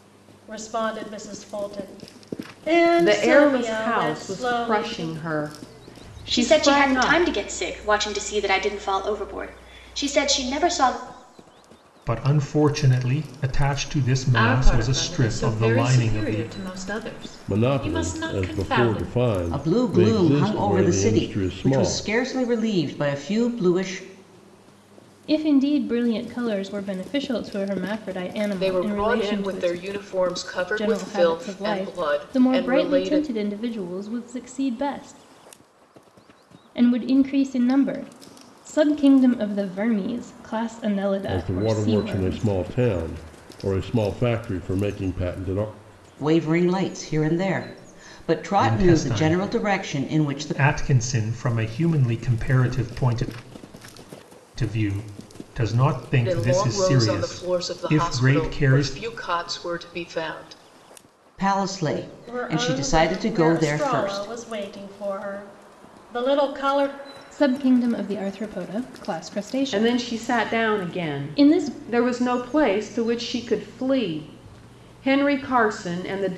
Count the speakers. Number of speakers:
9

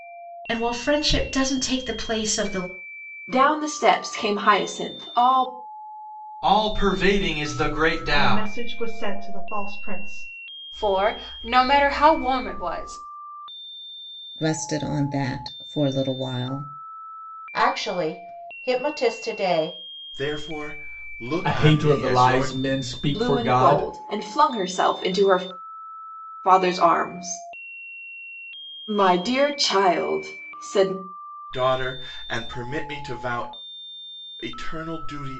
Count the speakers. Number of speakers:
9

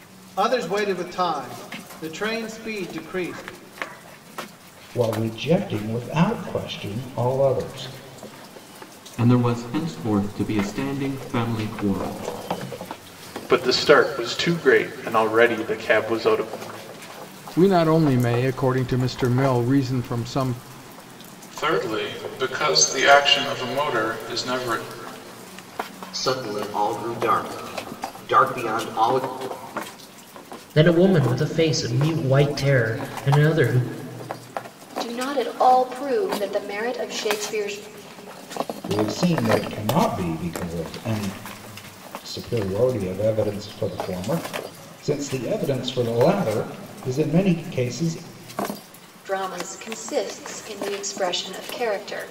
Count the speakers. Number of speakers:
9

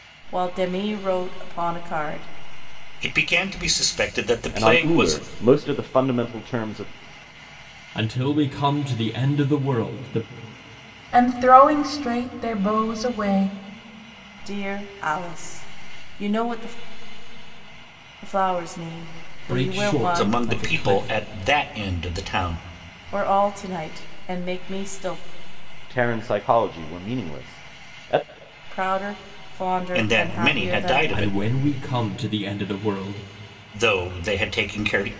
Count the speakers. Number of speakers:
5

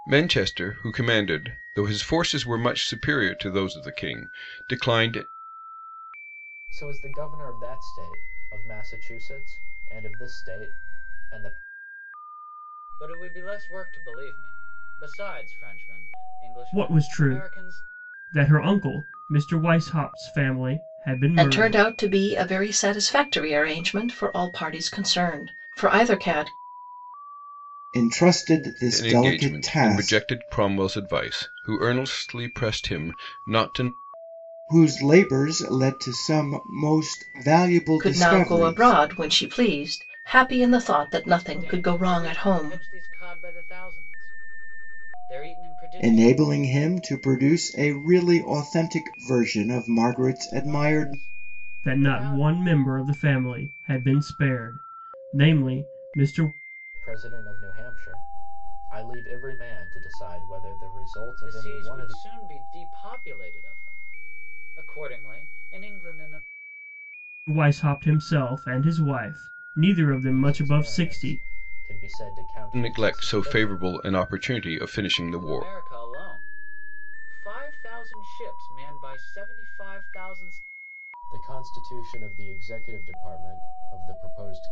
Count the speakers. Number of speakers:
6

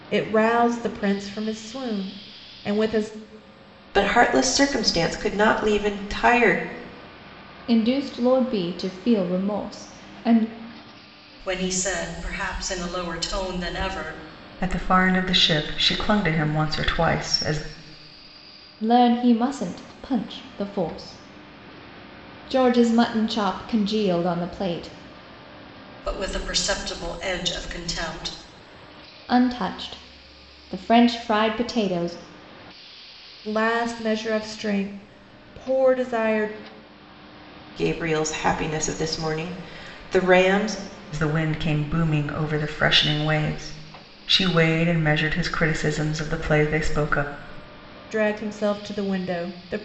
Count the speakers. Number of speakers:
5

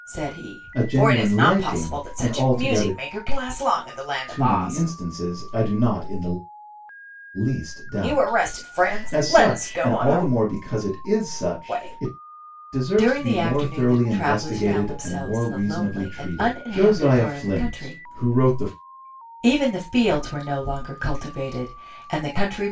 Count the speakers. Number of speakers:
2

